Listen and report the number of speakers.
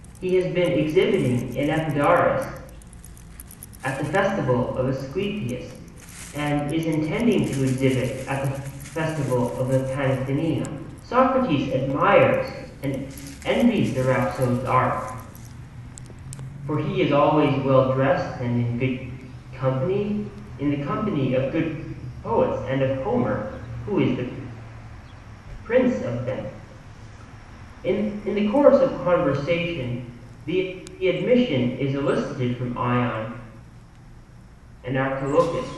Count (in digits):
1